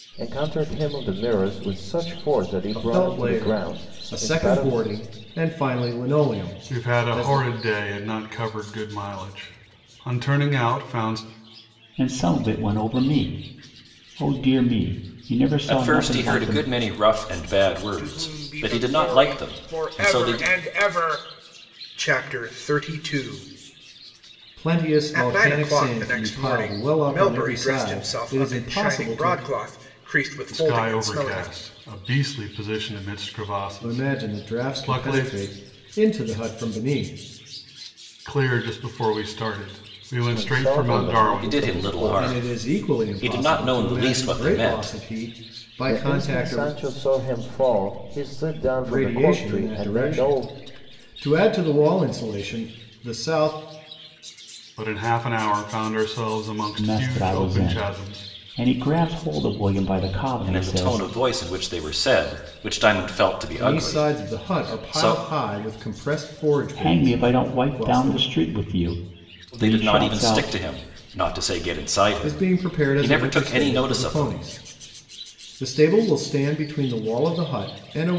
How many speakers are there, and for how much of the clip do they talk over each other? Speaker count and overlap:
6, about 38%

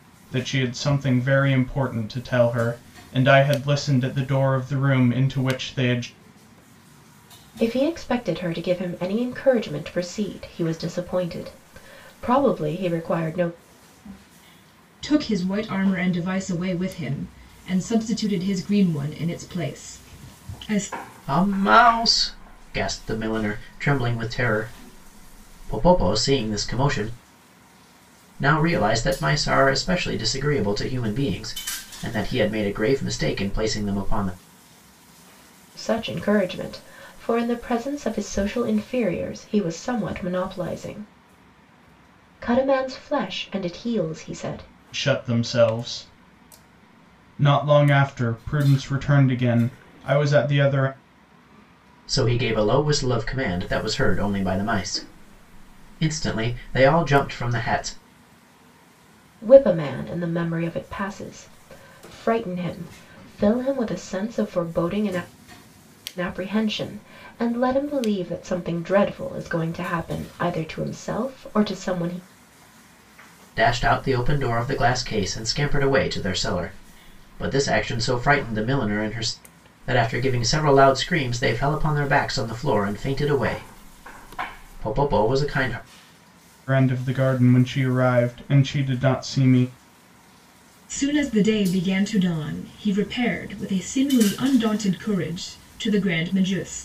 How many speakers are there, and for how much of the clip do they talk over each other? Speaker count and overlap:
4, no overlap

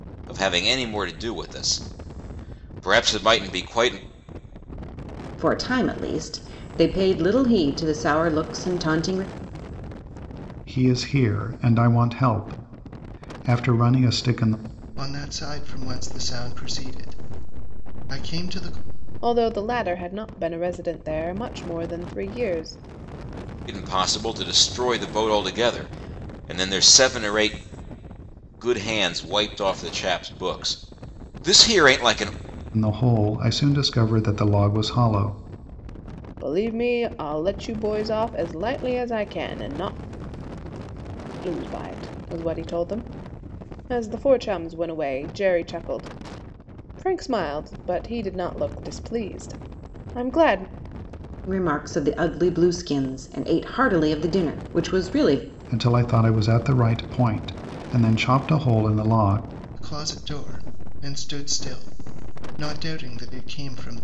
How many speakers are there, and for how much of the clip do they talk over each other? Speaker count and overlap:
5, no overlap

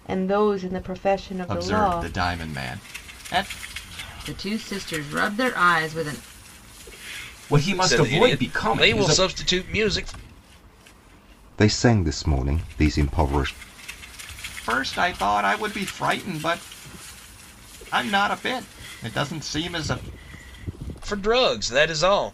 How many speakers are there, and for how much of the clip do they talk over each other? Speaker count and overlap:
6, about 9%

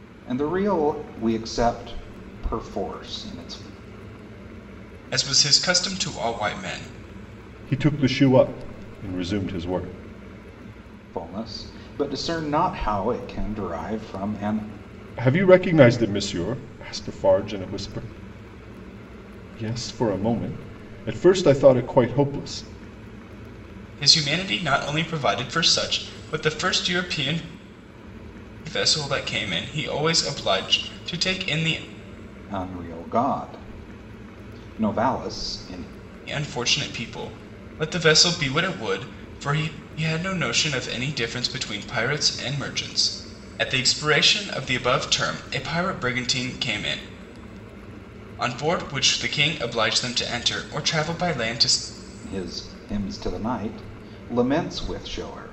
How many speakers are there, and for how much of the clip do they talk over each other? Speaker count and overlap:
3, no overlap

